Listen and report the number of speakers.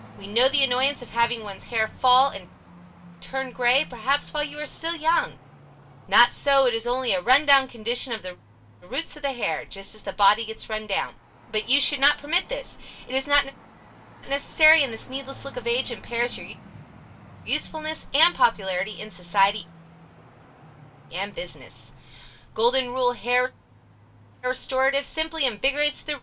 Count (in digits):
1